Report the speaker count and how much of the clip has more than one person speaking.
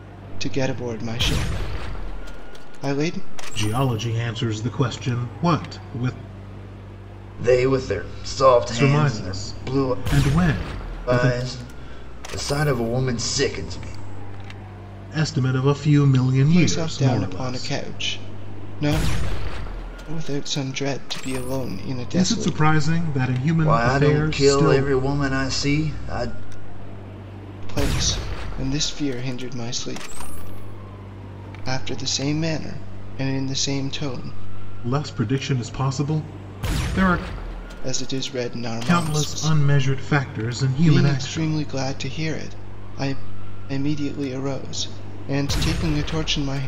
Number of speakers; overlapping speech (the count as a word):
three, about 13%